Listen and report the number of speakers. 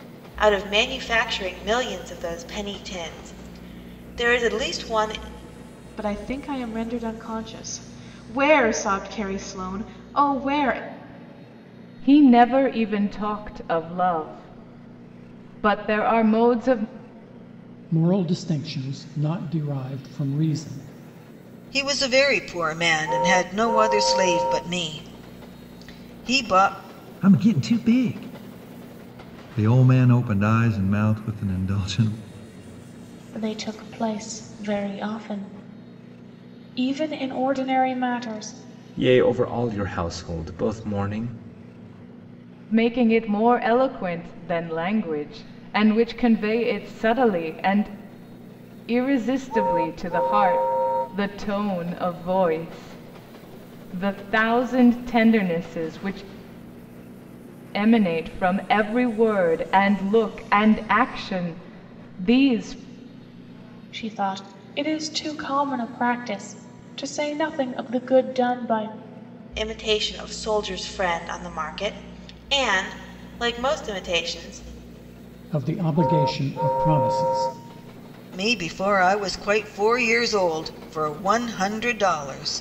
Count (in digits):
8